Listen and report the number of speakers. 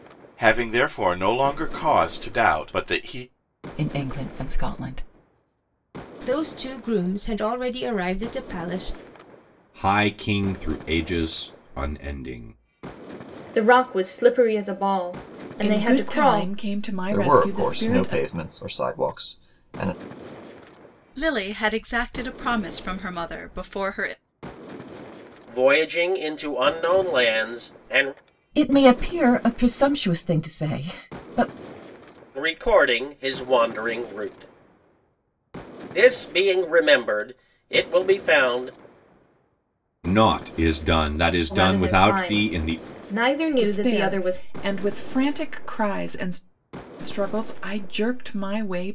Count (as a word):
ten